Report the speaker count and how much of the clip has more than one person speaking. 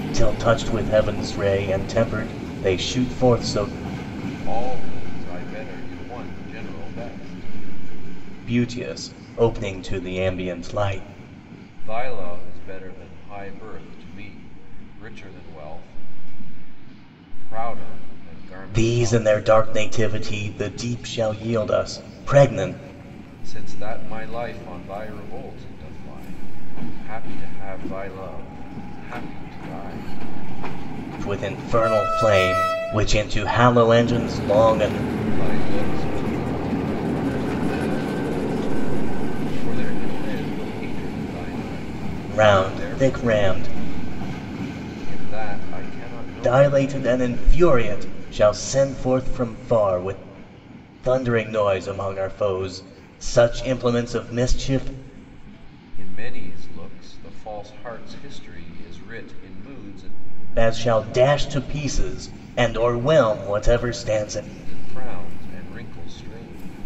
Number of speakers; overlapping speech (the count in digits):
2, about 5%